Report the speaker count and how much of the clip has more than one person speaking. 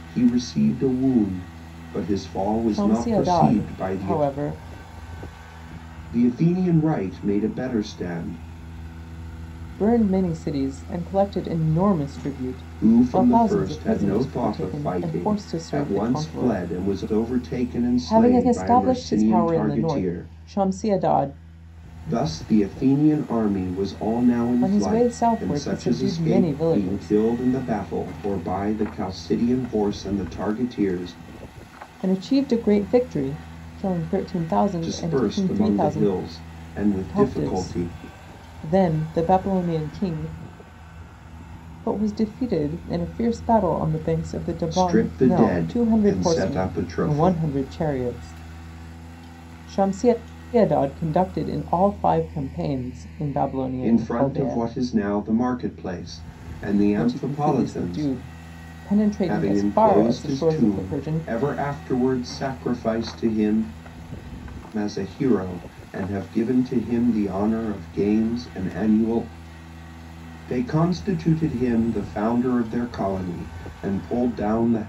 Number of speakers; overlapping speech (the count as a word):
two, about 28%